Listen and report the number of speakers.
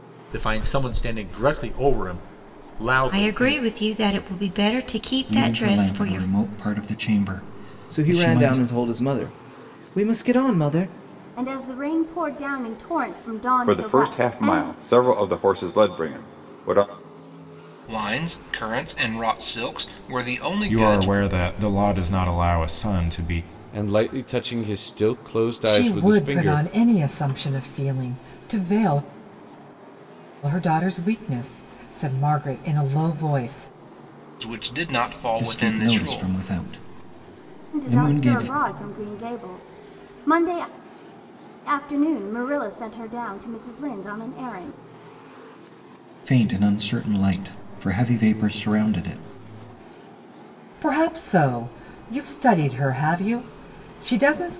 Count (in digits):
10